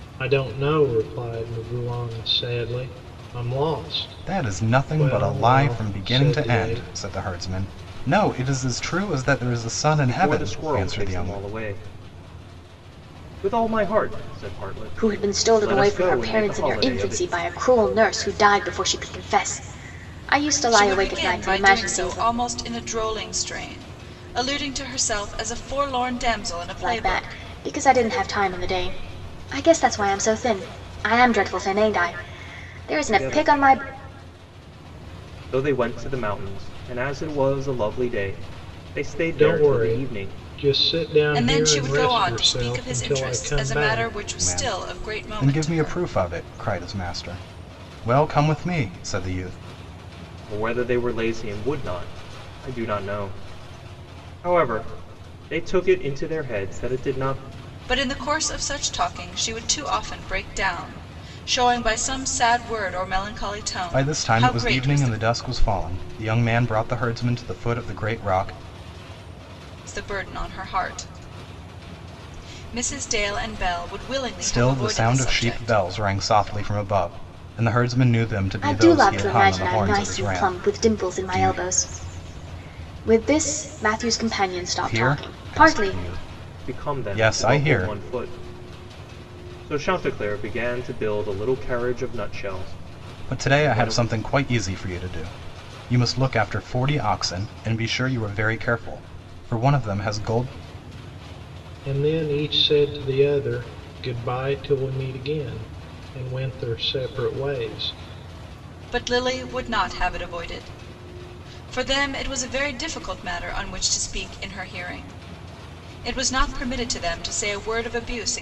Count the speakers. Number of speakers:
5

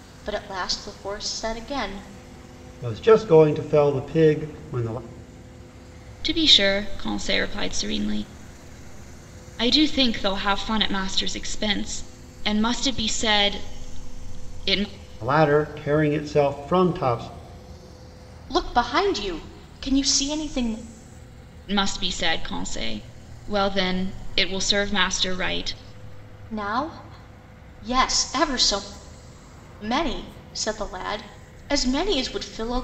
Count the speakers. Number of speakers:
3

